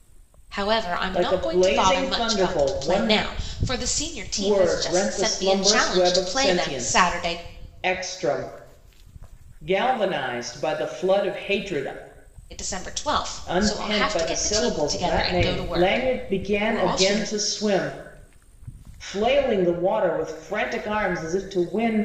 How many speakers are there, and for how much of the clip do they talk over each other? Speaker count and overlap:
2, about 41%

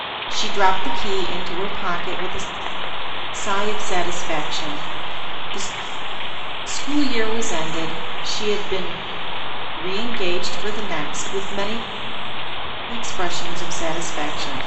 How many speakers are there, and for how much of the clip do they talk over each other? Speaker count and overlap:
1, no overlap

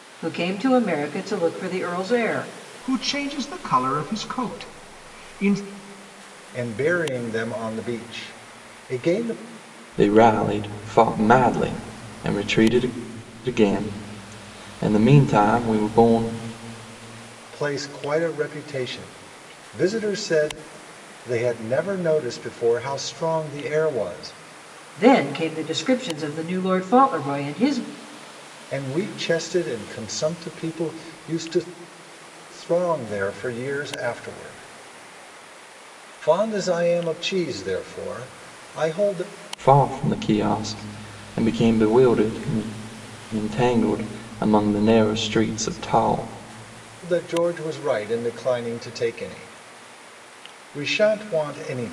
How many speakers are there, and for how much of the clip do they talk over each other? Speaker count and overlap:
4, no overlap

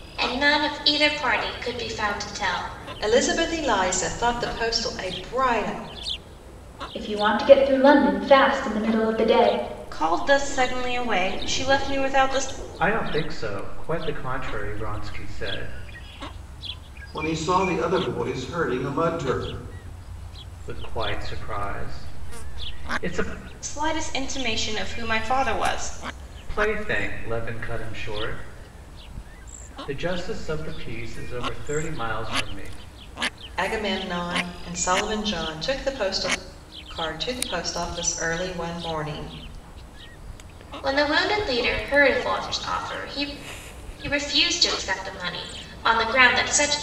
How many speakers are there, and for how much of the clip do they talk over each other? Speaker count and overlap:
6, no overlap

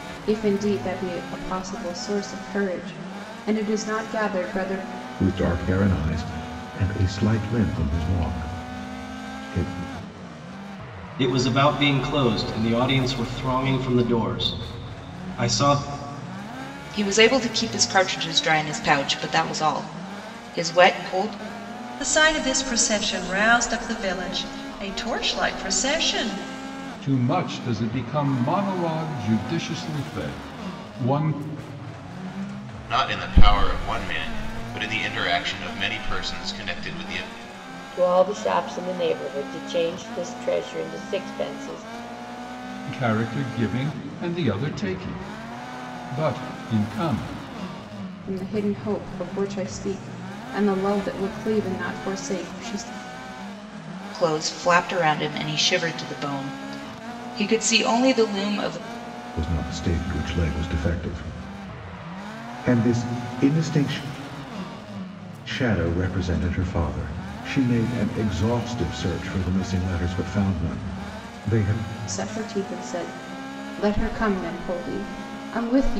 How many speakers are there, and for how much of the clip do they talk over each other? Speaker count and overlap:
8, no overlap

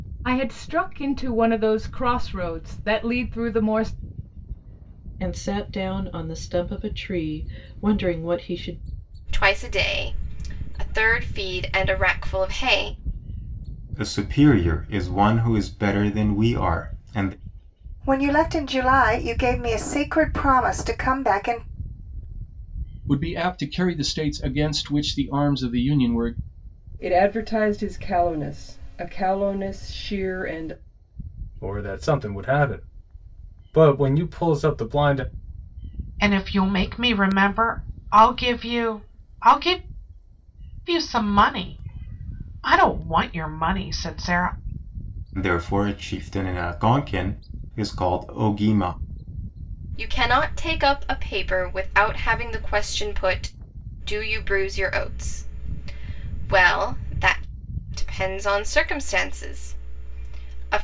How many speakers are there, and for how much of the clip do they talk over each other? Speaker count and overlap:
9, no overlap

